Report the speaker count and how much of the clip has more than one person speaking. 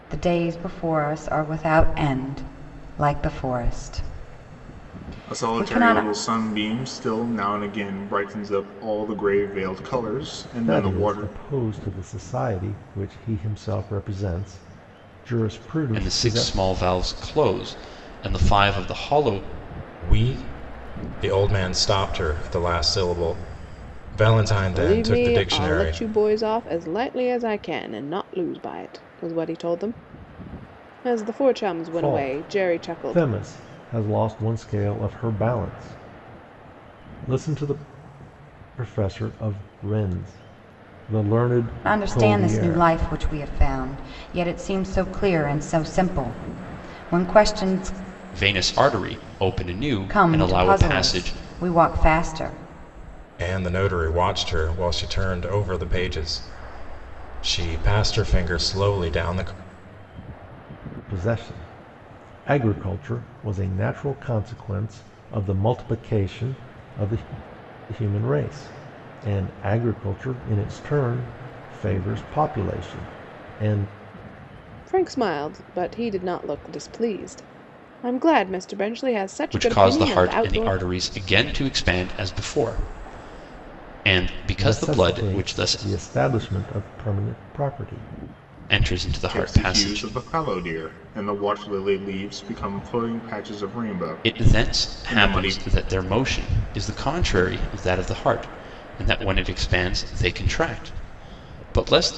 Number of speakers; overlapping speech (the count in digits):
6, about 12%